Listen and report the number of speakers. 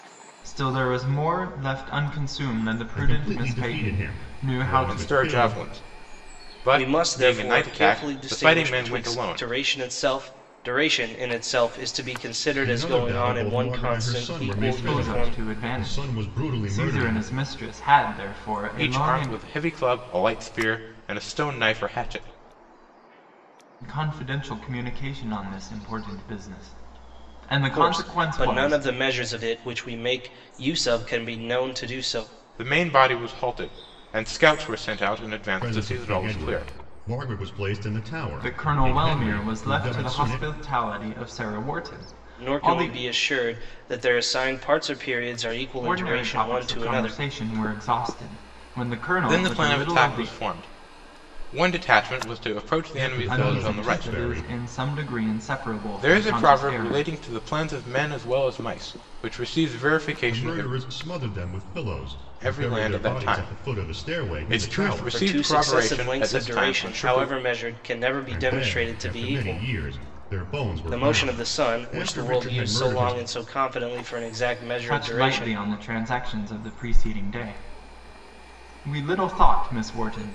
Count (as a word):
four